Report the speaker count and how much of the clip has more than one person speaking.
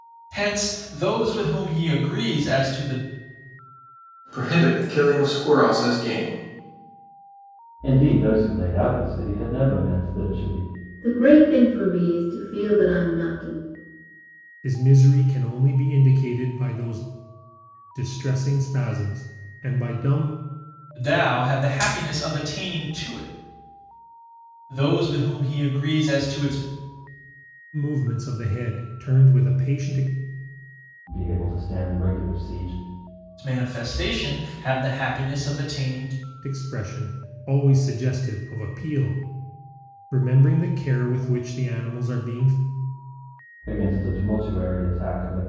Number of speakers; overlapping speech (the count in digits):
5, no overlap